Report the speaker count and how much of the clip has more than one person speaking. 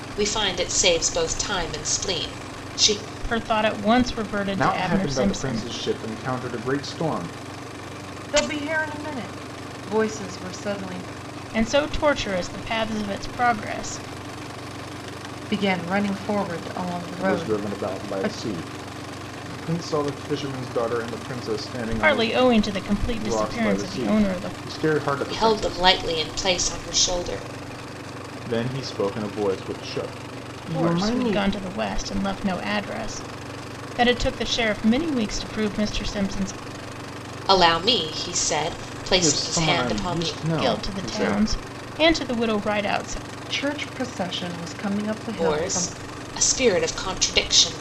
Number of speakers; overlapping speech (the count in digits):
4, about 17%